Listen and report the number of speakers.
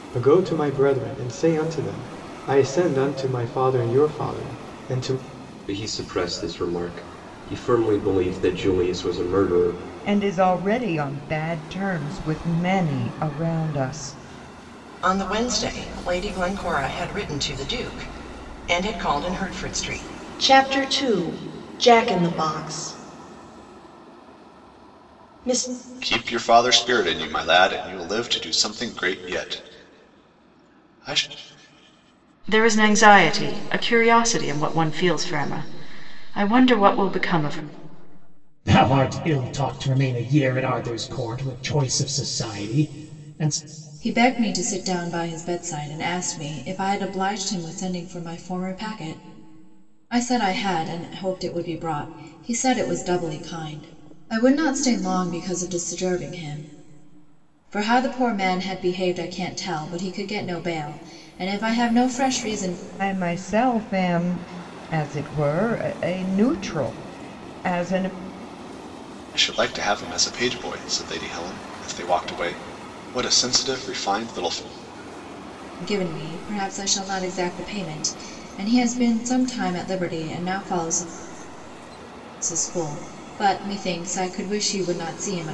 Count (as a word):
nine